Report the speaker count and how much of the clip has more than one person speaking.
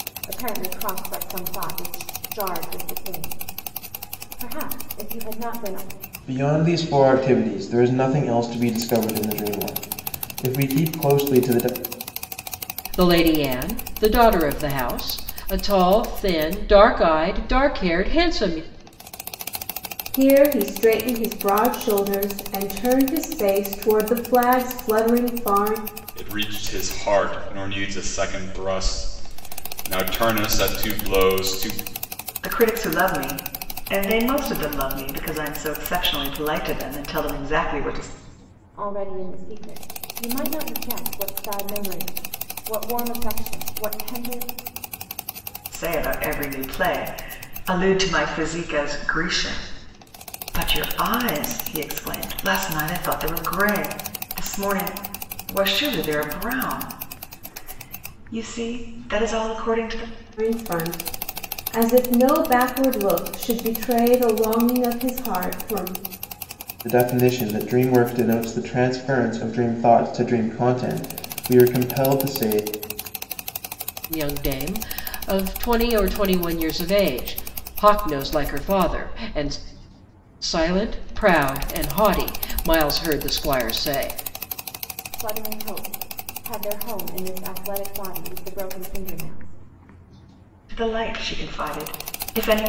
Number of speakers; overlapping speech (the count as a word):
six, no overlap